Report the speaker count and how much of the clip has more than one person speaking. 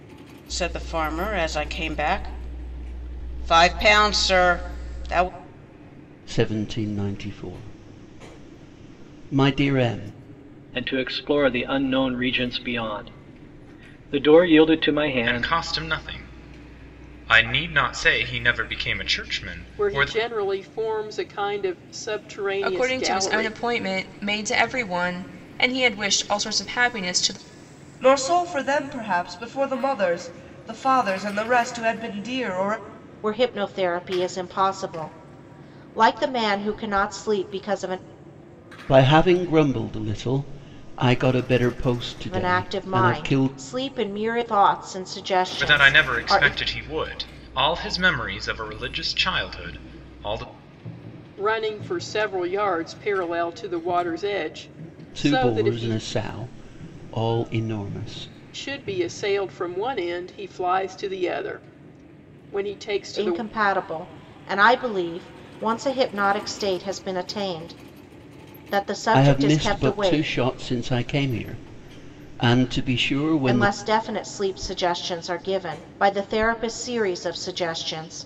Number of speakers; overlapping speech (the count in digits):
8, about 9%